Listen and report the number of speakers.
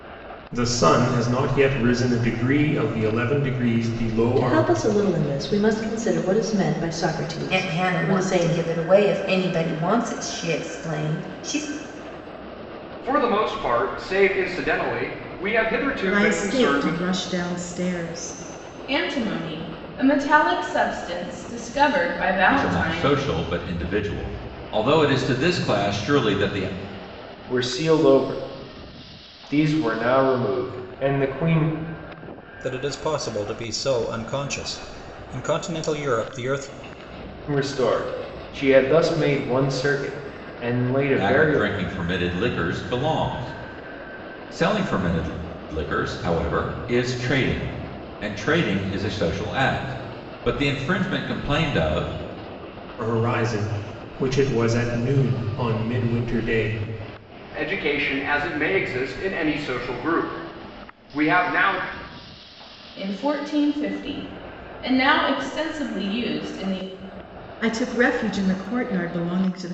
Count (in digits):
9